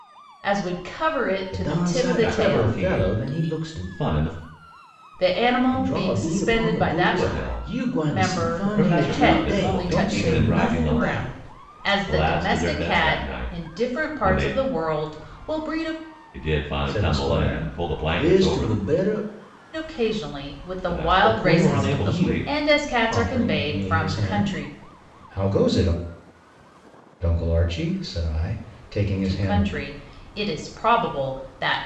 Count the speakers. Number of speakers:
three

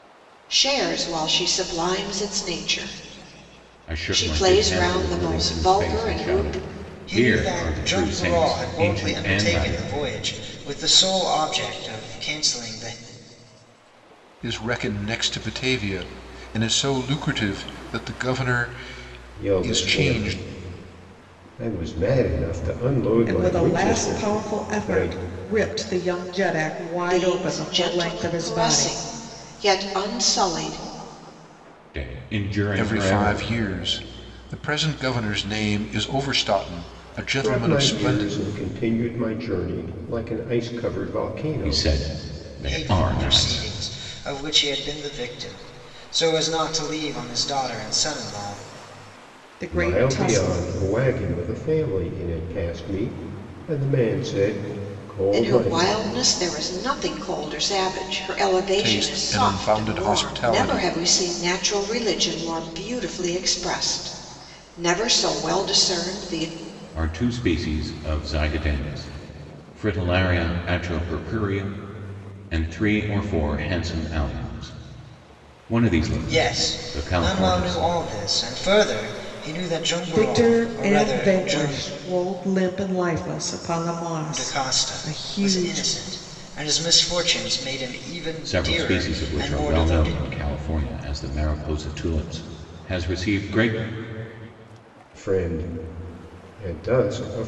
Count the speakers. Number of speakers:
six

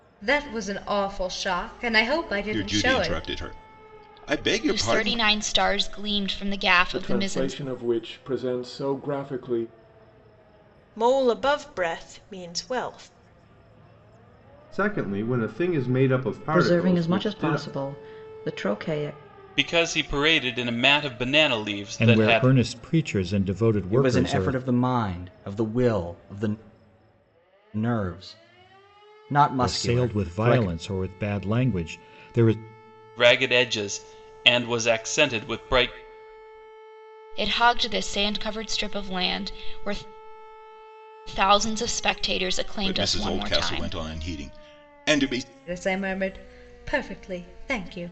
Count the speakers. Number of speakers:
ten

